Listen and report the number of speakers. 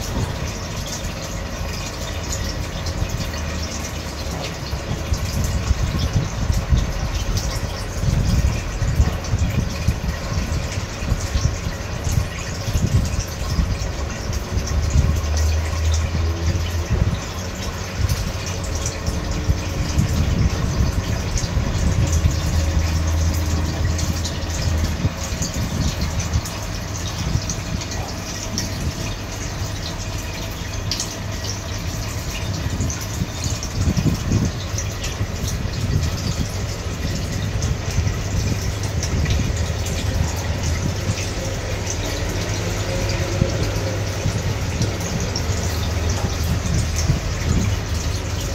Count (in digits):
0